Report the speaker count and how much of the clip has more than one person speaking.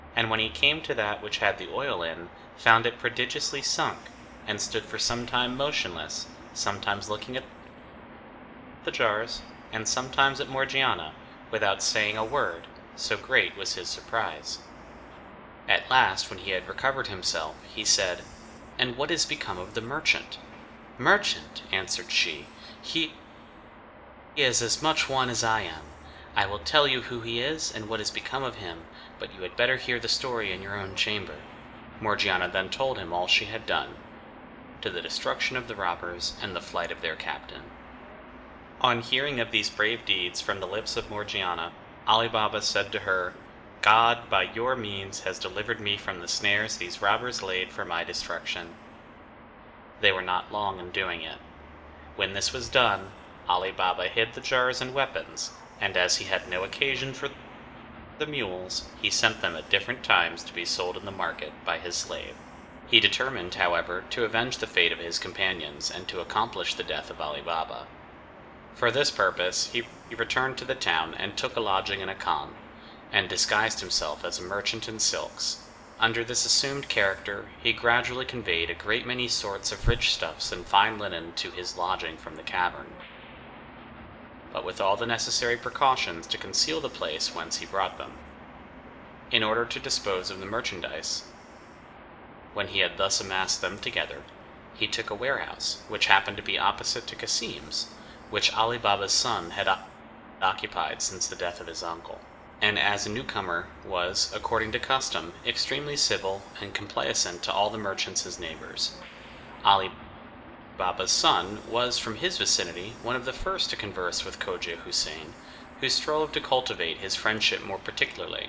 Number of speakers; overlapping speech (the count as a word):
one, no overlap